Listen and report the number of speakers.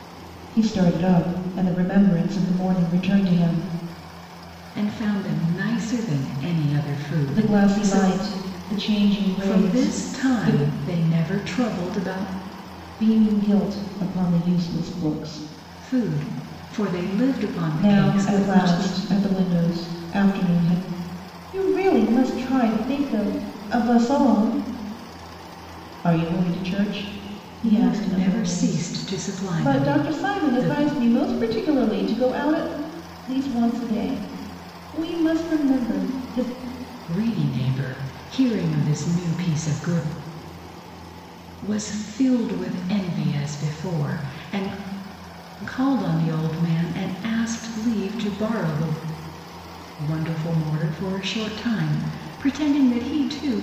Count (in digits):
2